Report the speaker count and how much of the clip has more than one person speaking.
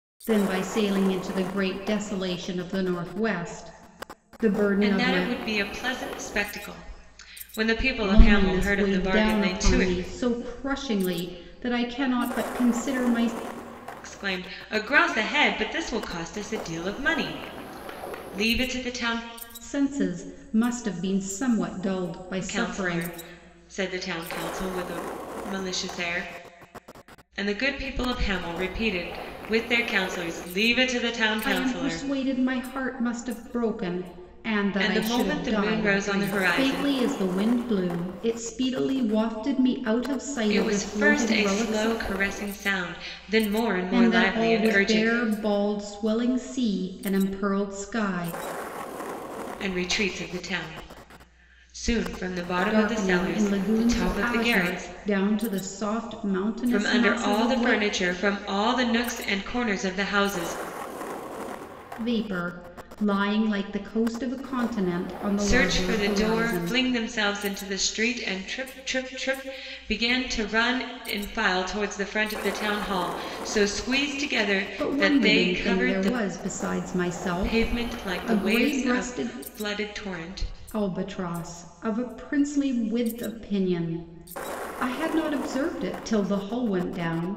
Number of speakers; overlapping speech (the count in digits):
2, about 20%